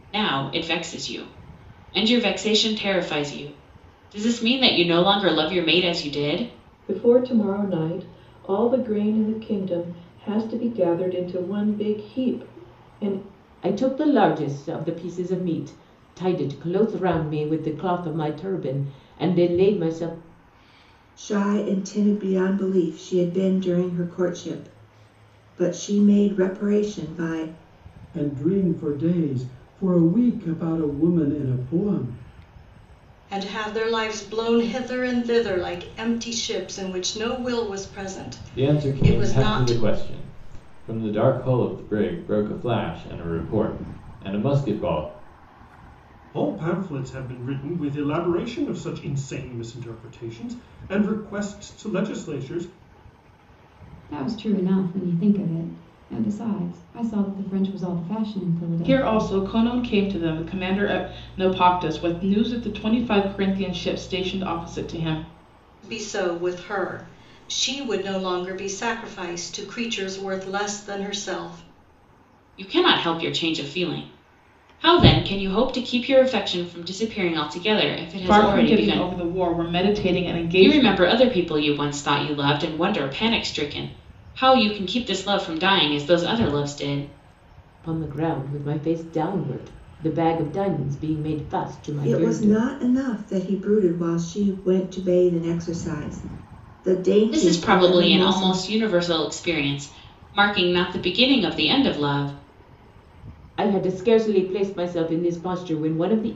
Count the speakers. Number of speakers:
ten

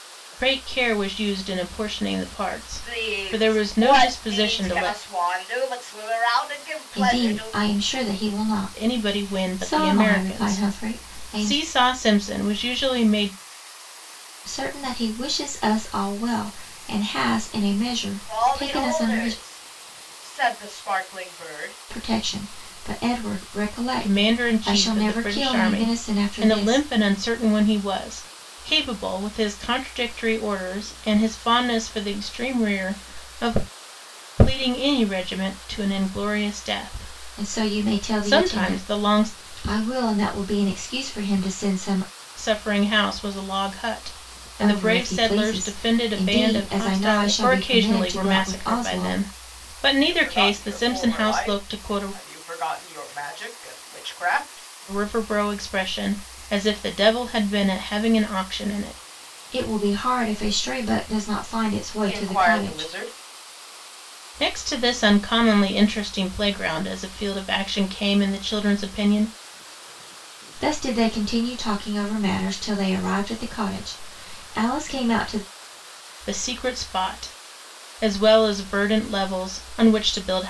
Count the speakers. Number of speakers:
three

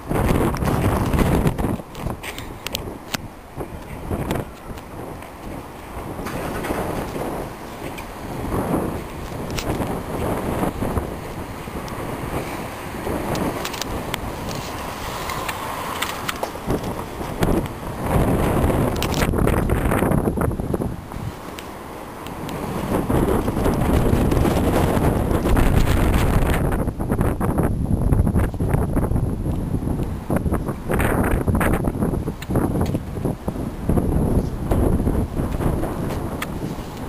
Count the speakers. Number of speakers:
zero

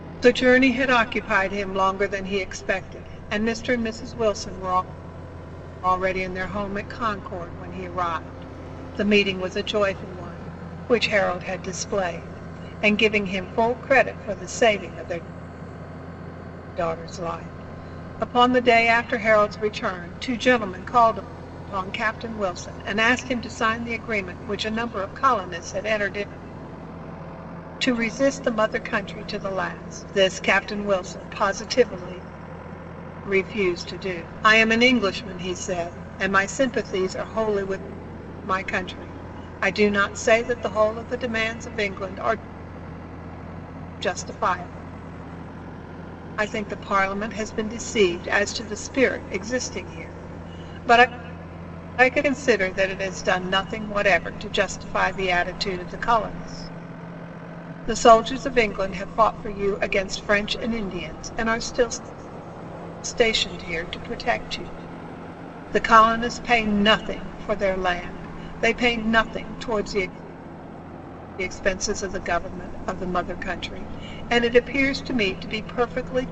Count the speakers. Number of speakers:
one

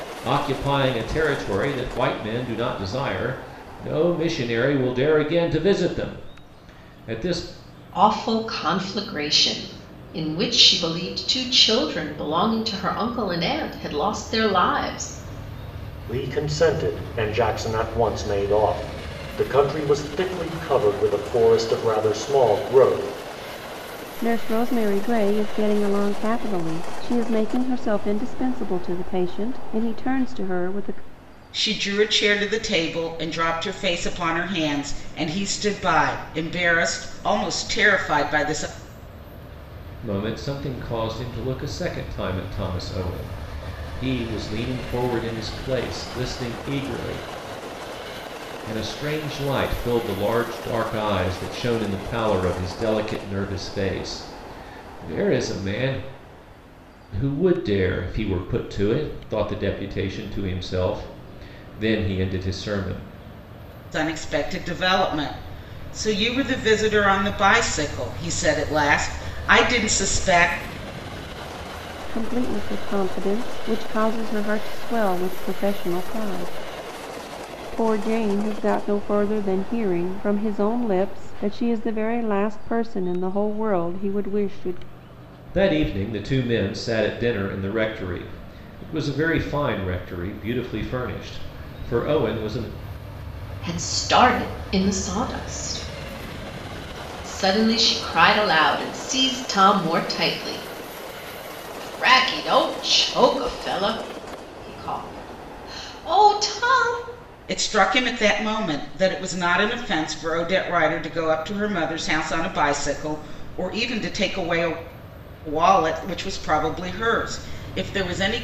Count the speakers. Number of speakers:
five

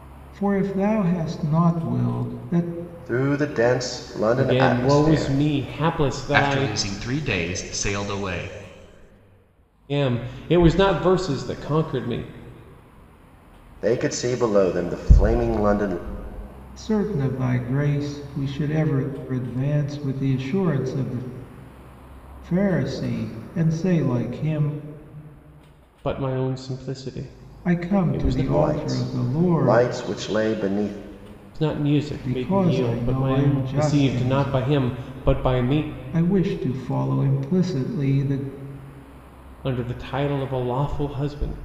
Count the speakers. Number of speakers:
four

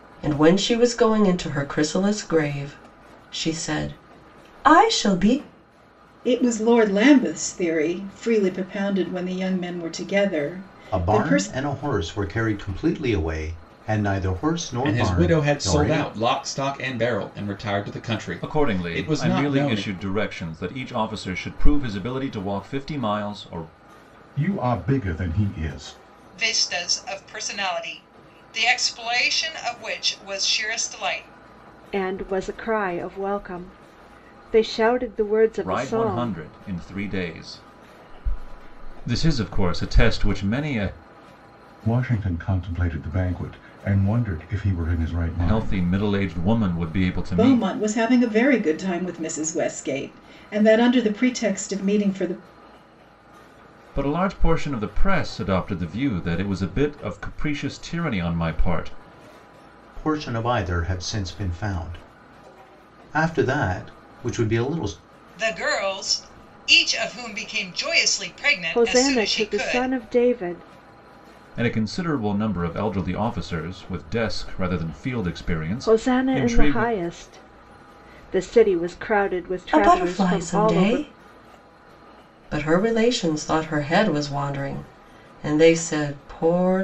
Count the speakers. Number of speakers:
eight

